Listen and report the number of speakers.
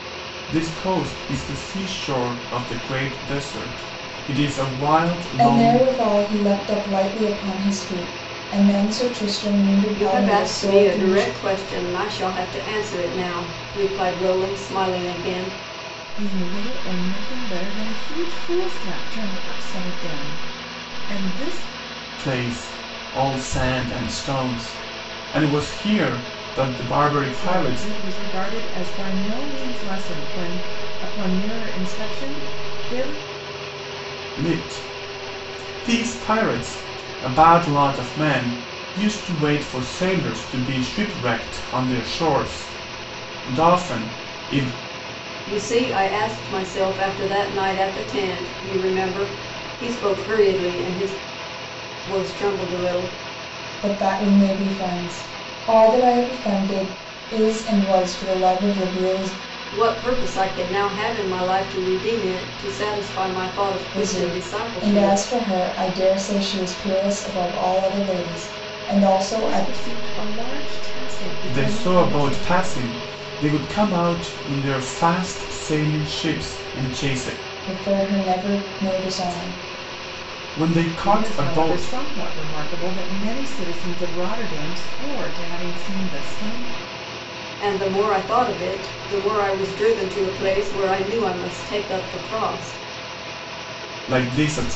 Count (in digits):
4